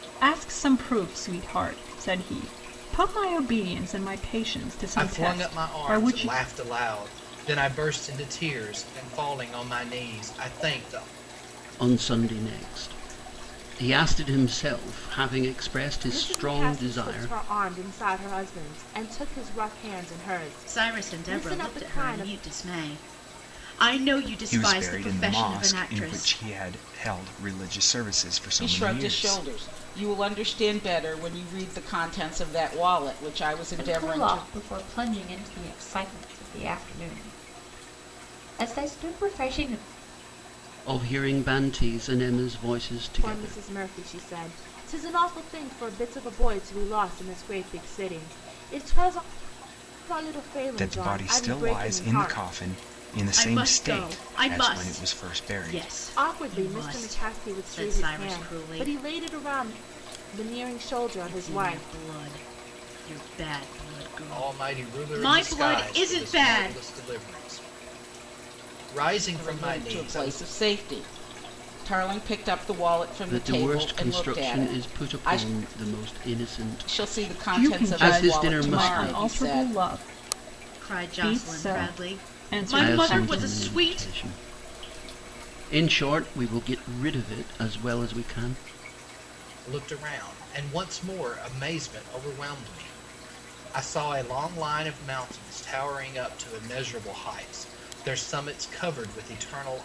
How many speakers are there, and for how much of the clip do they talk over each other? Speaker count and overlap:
8, about 28%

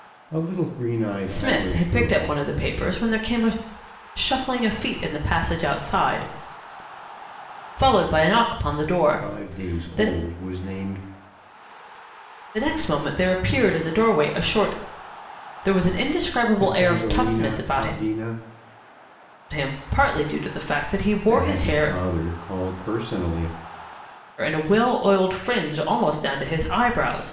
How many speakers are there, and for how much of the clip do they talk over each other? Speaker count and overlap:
2, about 16%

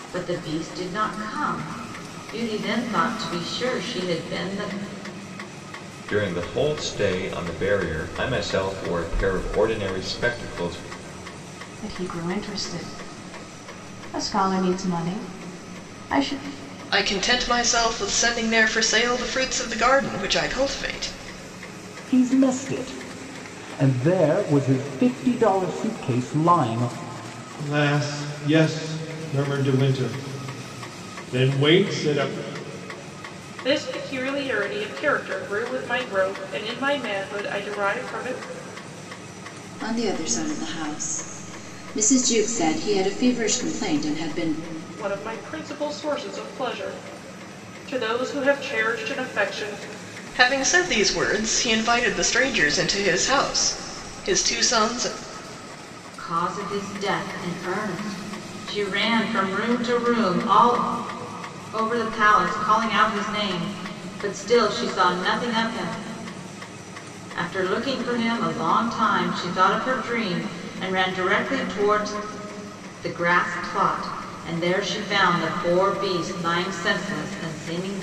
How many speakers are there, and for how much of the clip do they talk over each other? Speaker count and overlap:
8, no overlap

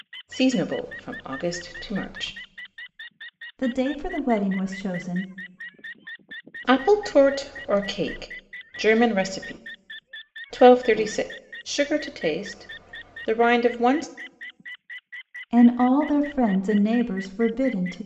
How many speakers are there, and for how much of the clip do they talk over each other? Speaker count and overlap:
2, no overlap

